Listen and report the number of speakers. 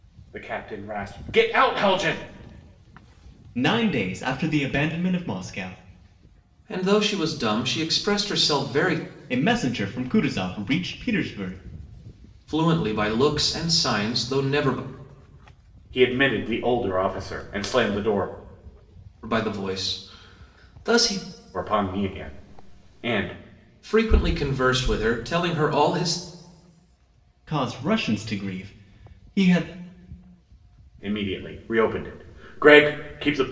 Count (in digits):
3